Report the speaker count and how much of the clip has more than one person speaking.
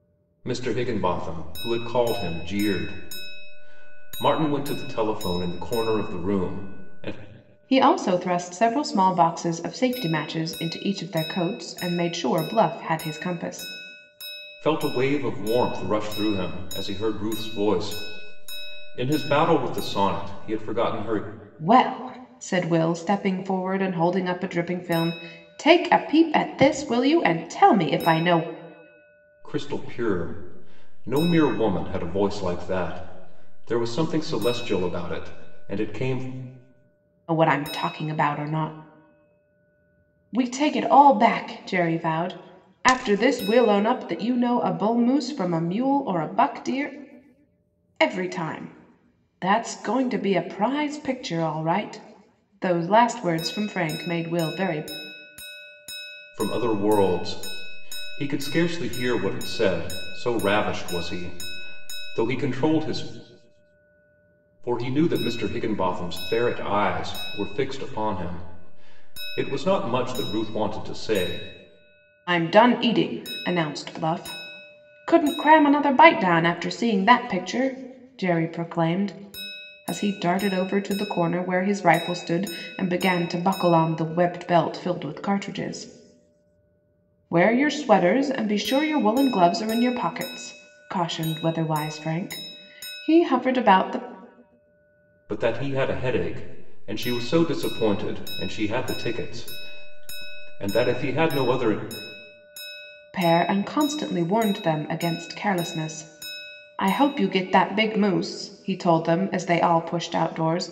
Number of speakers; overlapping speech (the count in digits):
2, no overlap